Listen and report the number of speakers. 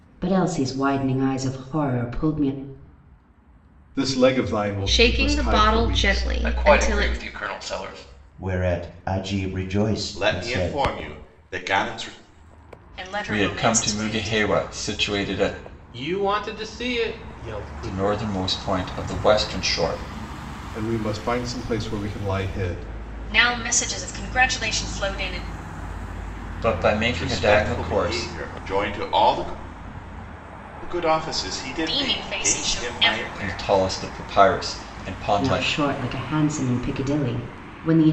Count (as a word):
nine